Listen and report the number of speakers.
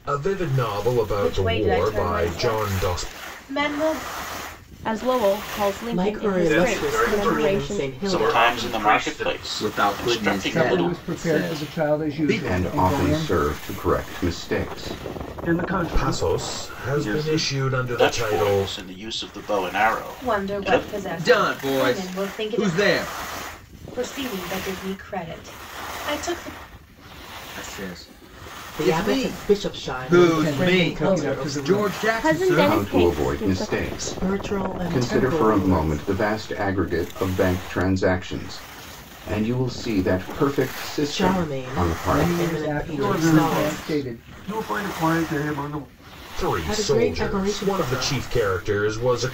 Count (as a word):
ten